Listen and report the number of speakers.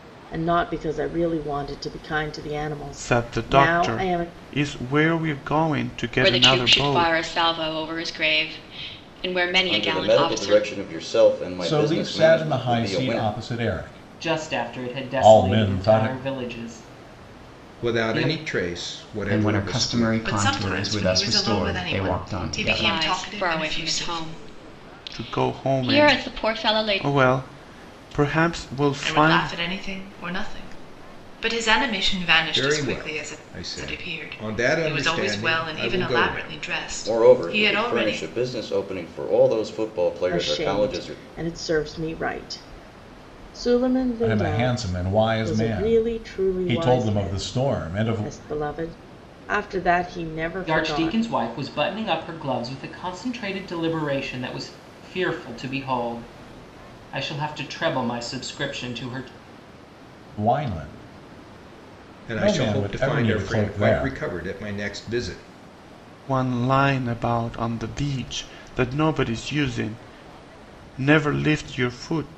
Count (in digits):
9